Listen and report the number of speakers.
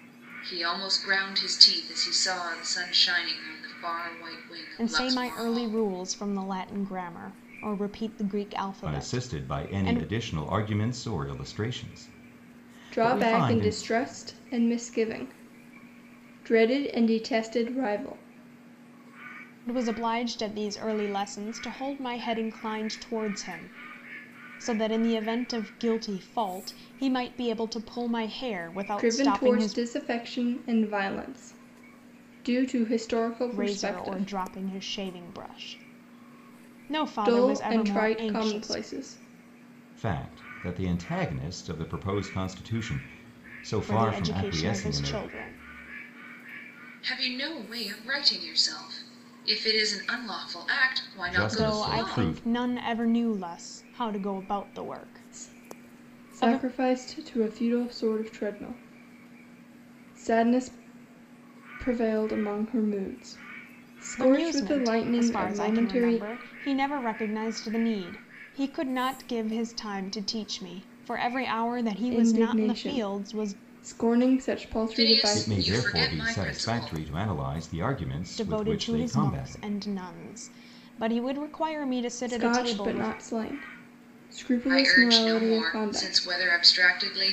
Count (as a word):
four